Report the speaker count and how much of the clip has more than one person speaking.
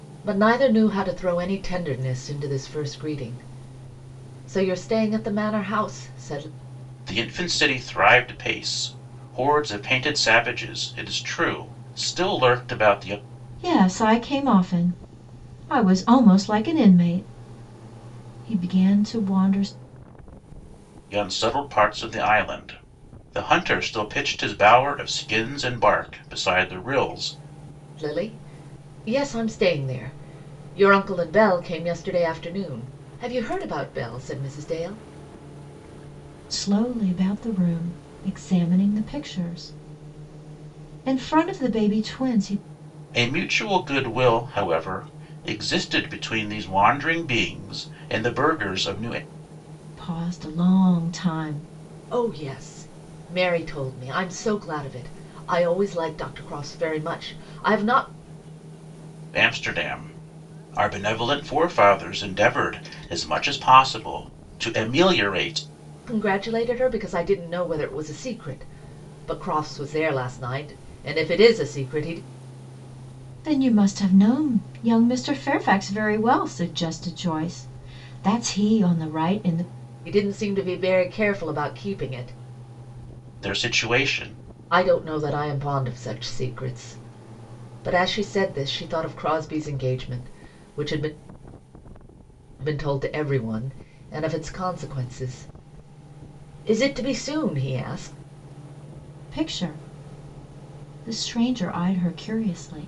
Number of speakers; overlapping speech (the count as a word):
three, no overlap